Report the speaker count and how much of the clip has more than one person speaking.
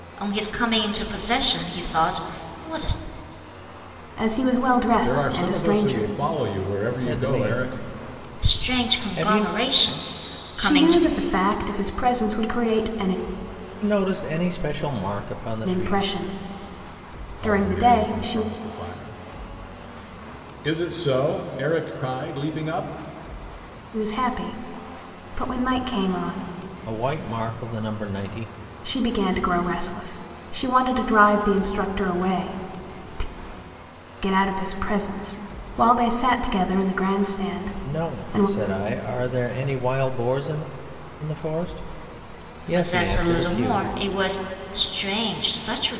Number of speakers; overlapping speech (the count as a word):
four, about 16%